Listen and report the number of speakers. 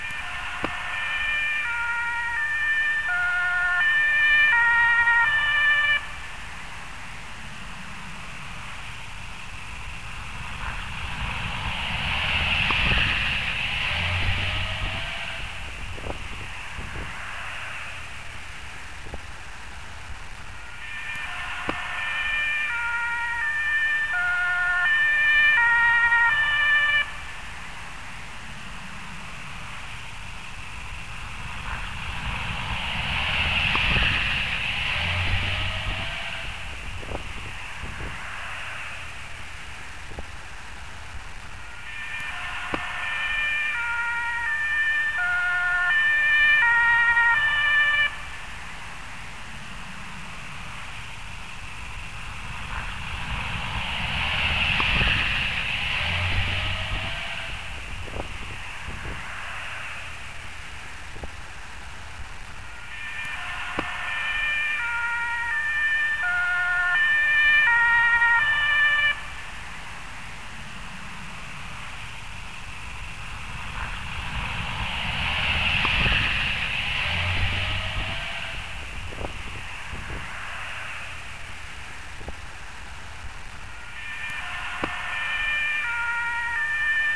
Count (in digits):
0